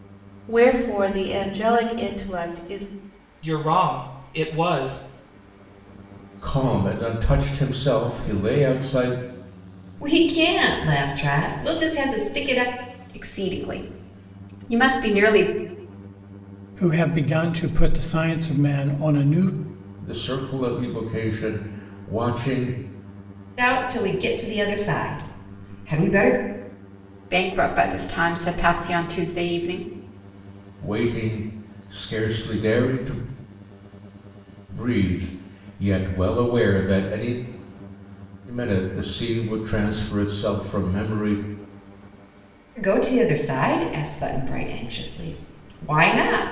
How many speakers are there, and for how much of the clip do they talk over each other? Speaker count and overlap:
6, no overlap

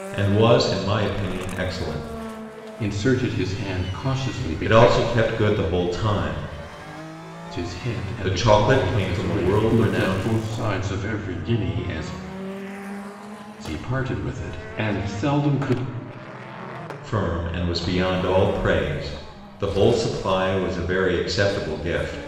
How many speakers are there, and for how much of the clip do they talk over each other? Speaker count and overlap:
2, about 12%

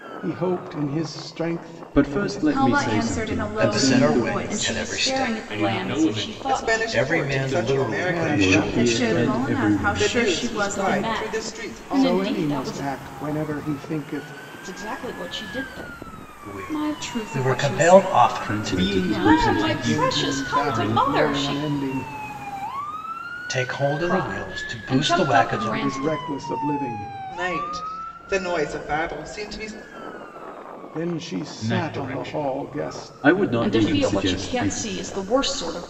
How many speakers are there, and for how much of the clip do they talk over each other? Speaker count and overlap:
7, about 60%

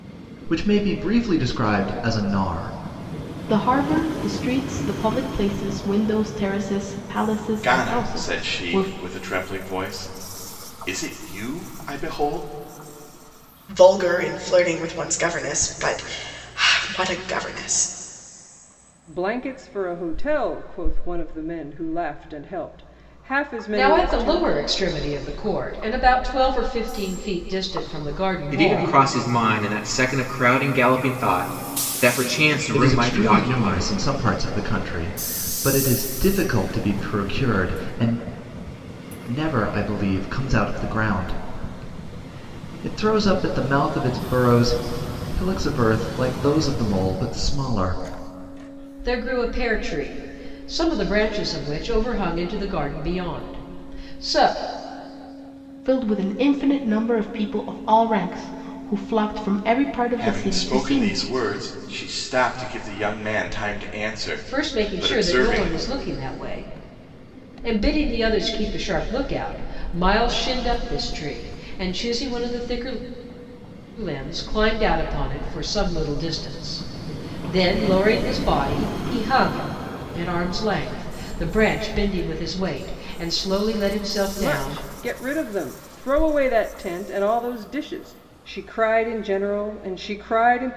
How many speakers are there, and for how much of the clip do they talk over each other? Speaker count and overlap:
7, about 7%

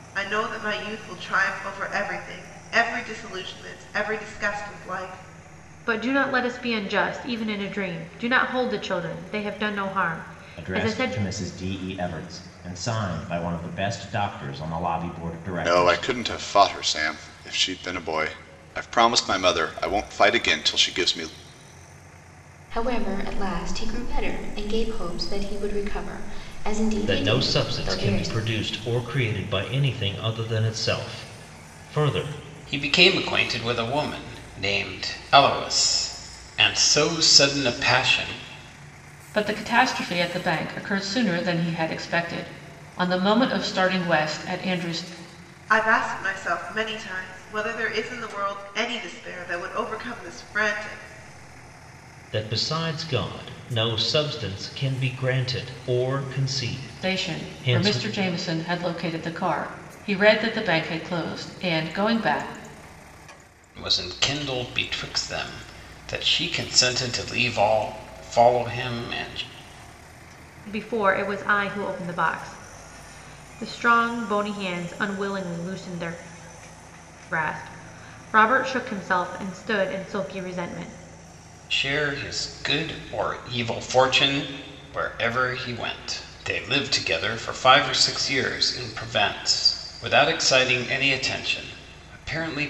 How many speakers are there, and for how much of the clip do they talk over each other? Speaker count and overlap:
8, about 4%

